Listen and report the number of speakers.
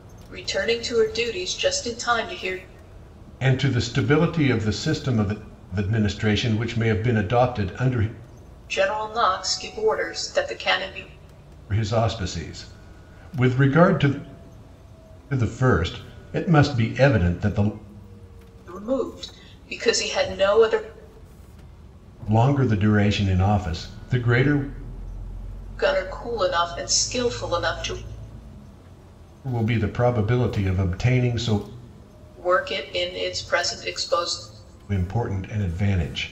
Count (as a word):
two